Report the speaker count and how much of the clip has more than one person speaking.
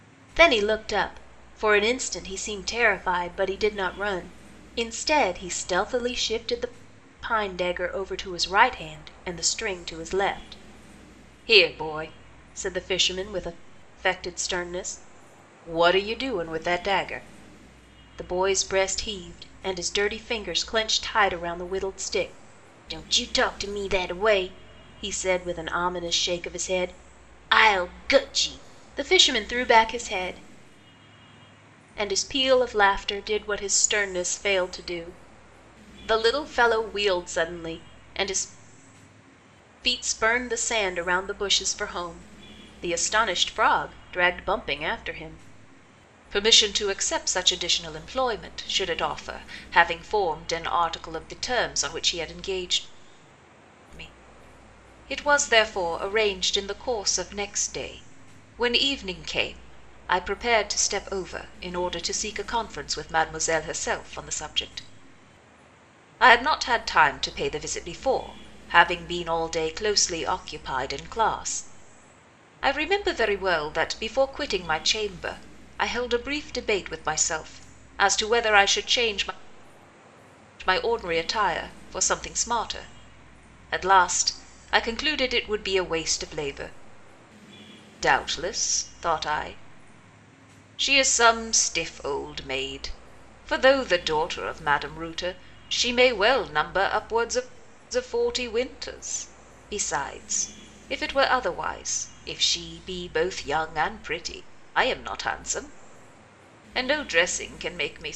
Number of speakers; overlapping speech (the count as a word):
one, no overlap